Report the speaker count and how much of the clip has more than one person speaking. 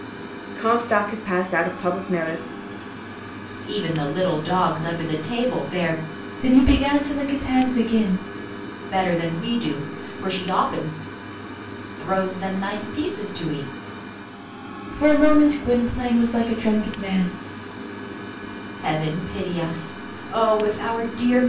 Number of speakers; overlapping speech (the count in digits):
3, no overlap